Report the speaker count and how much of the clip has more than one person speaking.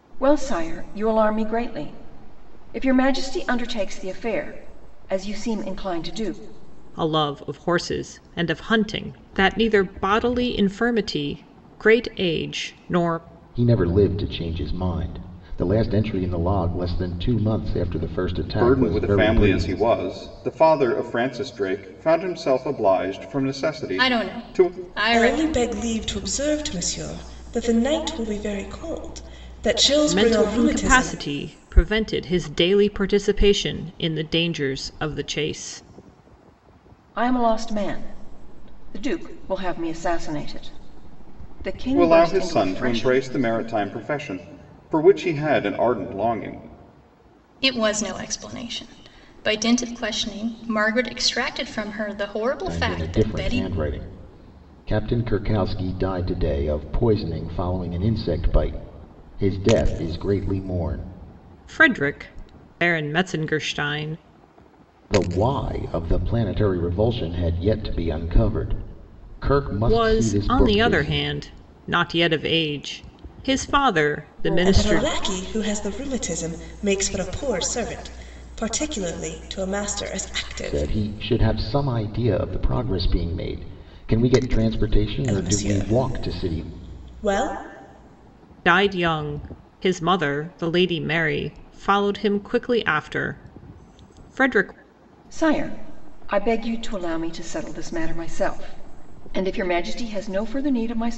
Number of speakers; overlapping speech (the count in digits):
6, about 10%